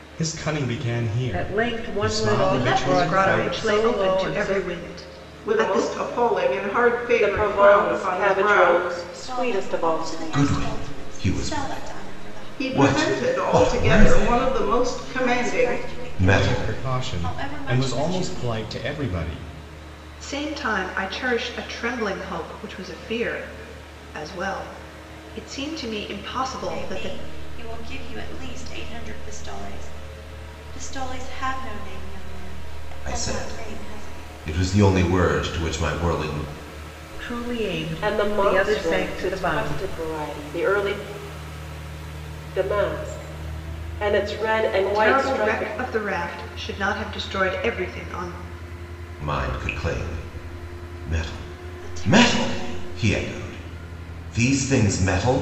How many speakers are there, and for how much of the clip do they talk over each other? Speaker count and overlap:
7, about 36%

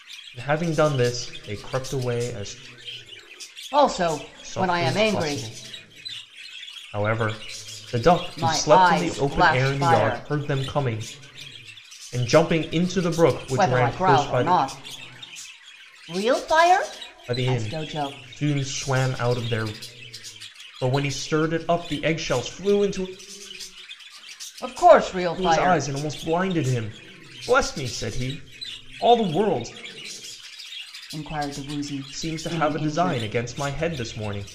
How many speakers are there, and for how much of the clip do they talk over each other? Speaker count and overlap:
2, about 19%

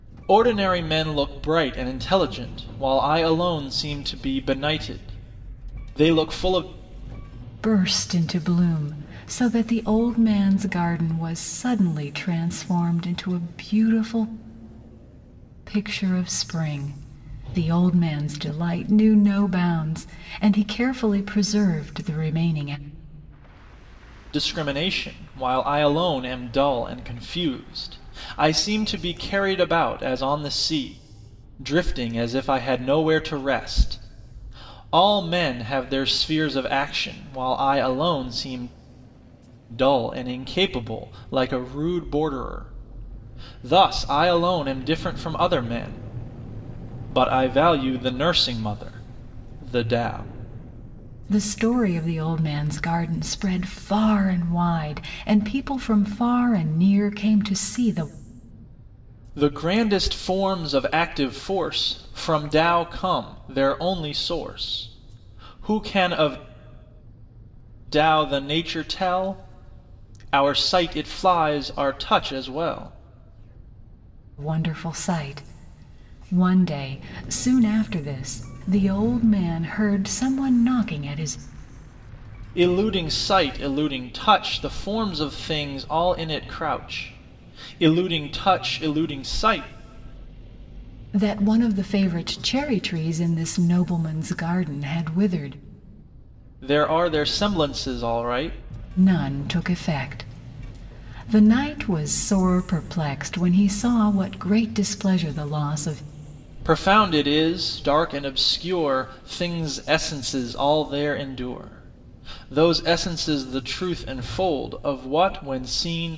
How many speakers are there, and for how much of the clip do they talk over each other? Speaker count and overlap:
2, no overlap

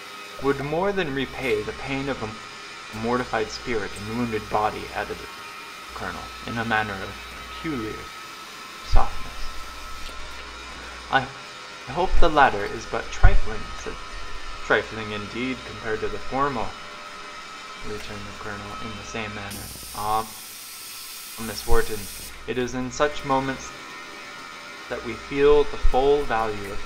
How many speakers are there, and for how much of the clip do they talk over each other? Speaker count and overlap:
1, no overlap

